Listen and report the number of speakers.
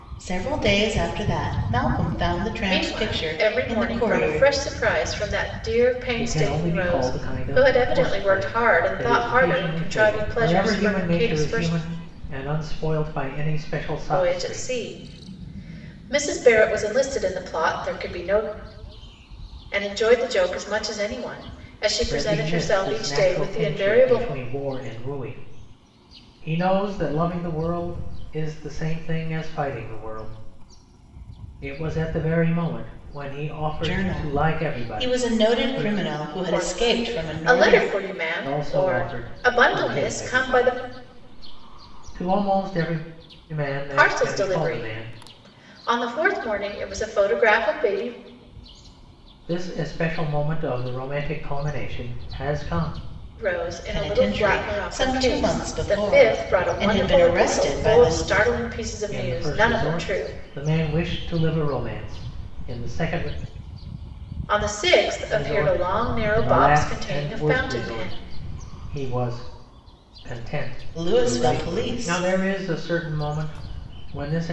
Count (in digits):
3